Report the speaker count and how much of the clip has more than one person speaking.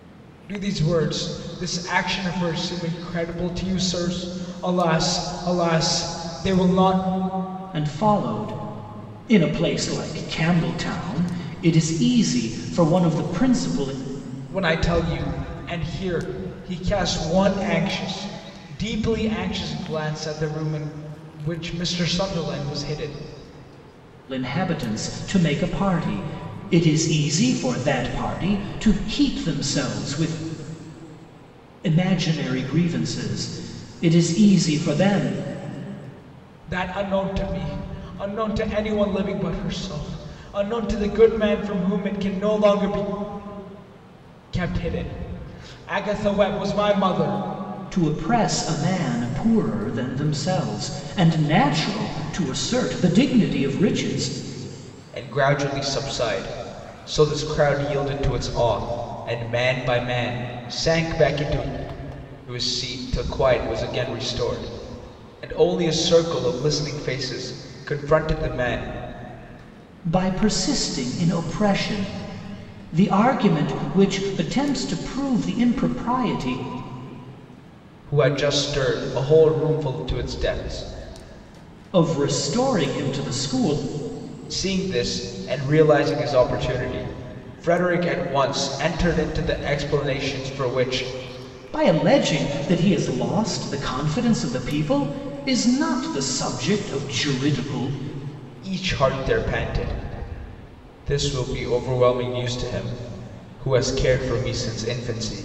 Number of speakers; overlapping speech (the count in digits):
2, no overlap